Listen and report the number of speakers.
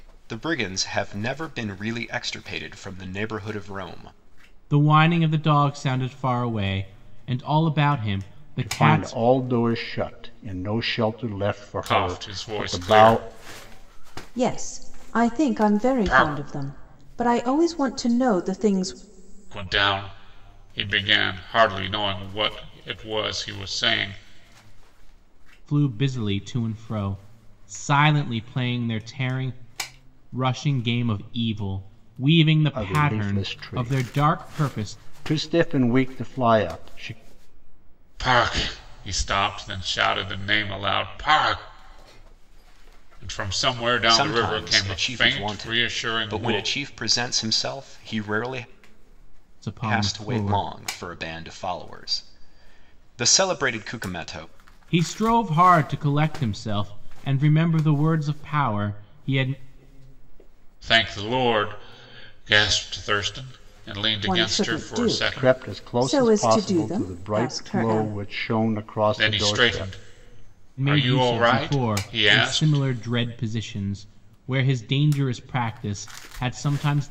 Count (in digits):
5